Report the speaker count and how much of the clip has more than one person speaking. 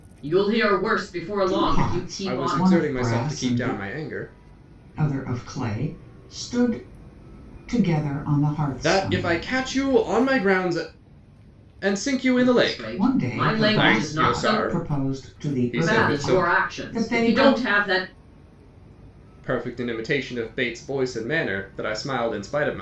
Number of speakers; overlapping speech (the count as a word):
three, about 36%